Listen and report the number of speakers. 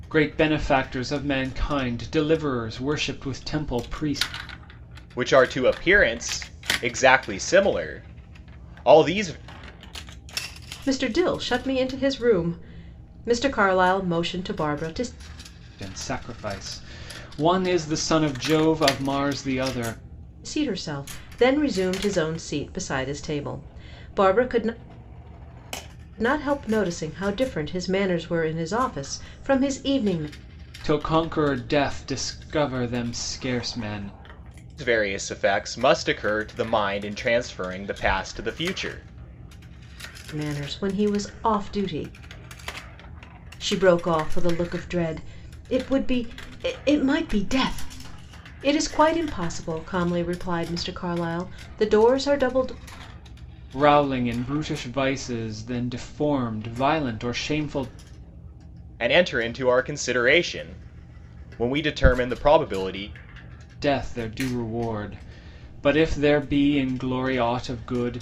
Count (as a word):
three